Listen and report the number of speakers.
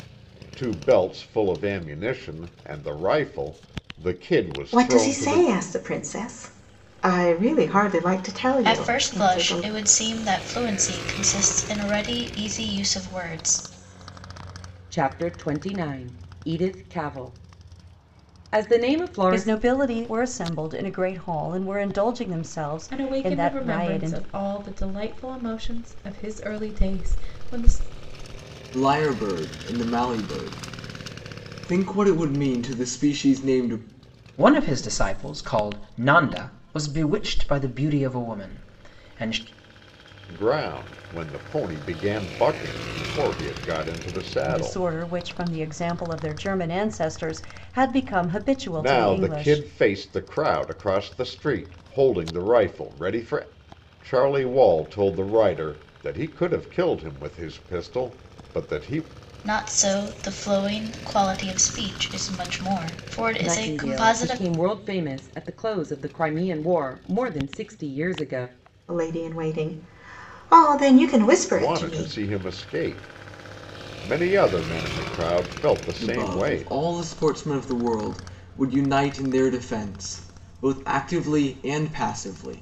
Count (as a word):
eight